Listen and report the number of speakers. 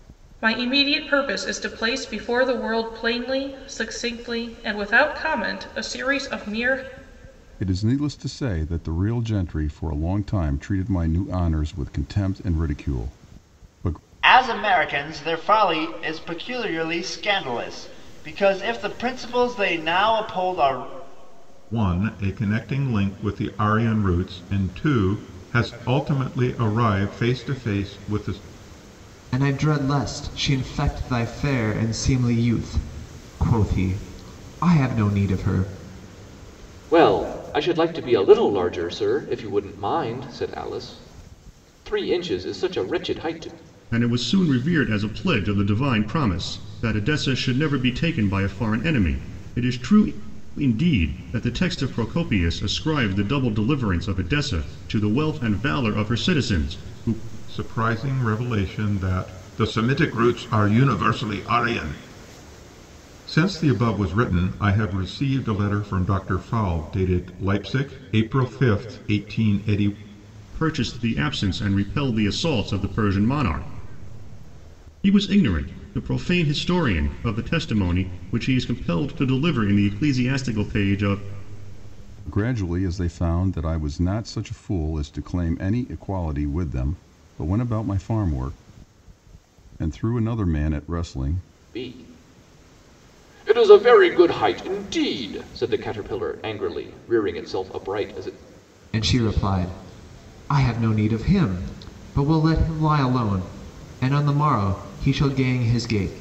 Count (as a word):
seven